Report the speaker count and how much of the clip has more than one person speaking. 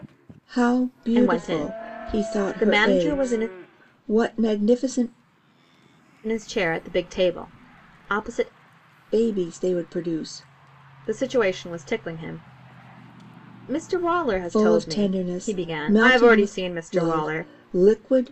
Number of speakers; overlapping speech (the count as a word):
two, about 29%